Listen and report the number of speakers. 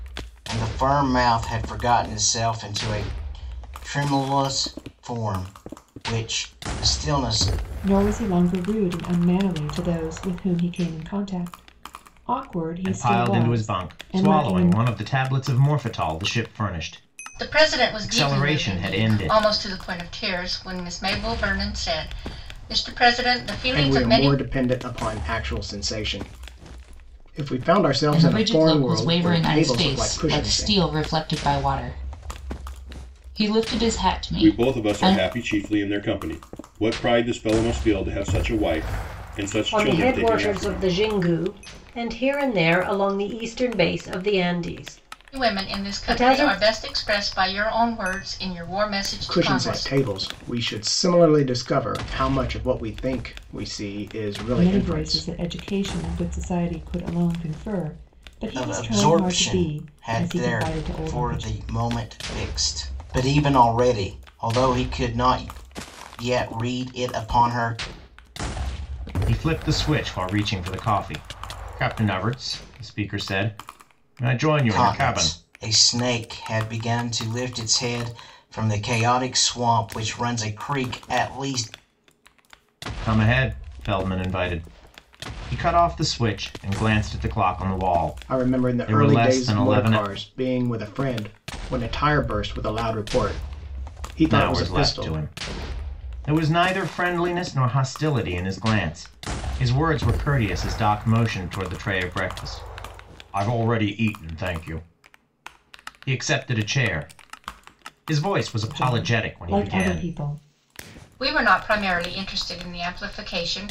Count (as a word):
eight